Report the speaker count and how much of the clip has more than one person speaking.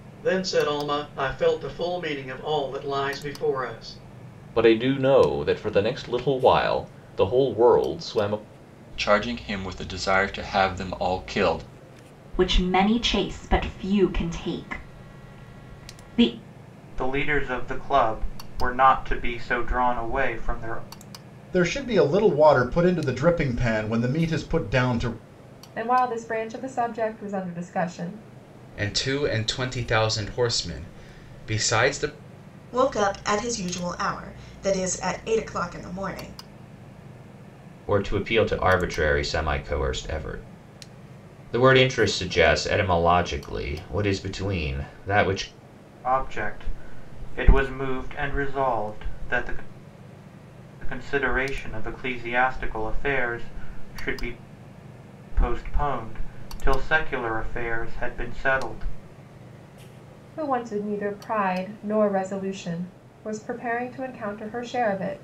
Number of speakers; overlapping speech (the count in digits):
10, no overlap